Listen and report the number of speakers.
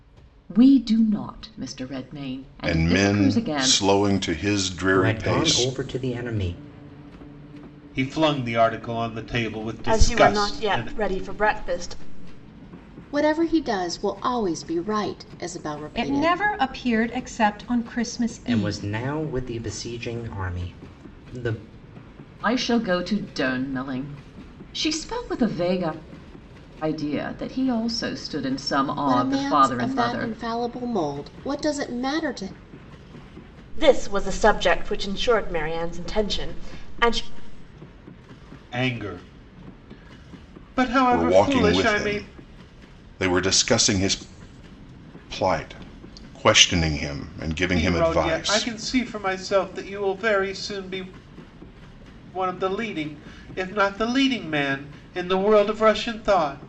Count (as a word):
seven